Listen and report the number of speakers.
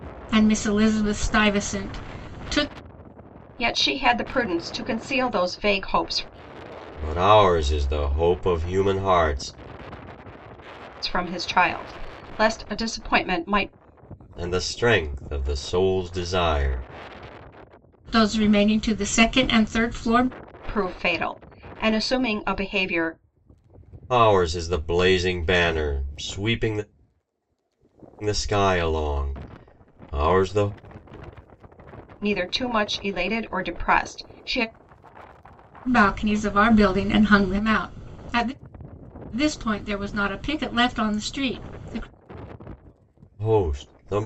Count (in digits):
3